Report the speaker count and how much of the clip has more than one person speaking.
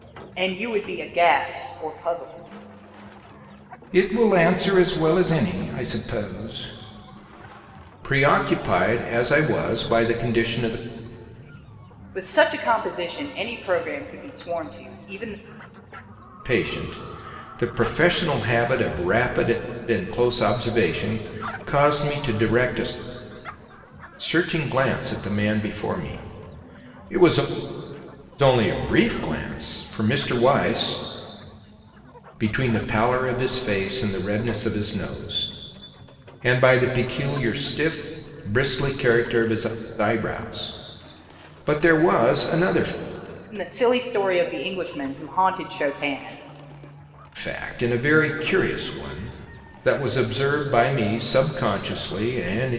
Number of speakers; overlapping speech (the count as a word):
two, no overlap